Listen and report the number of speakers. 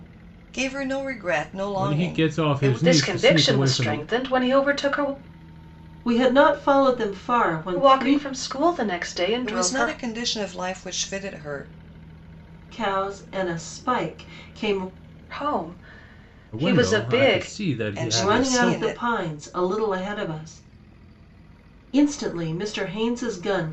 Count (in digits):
4